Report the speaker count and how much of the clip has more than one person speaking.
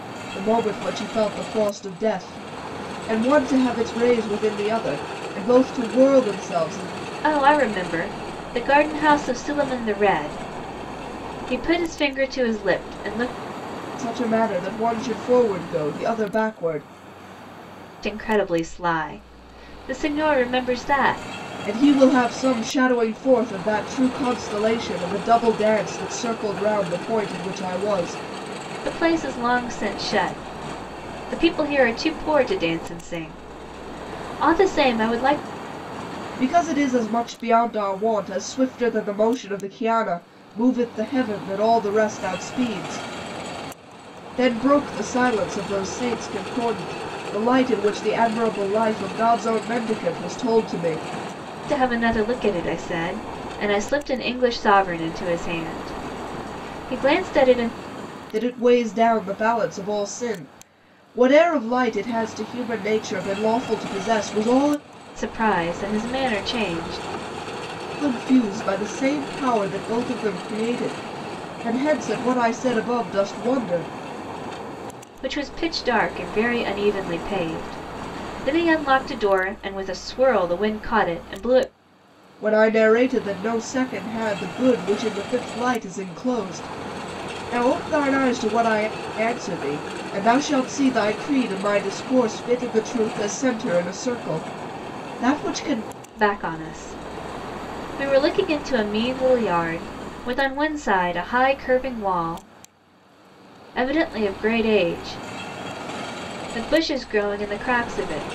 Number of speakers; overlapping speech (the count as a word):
two, no overlap